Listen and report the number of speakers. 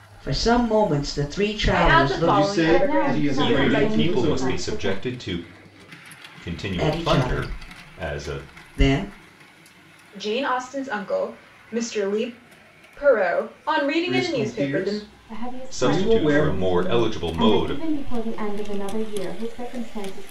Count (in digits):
5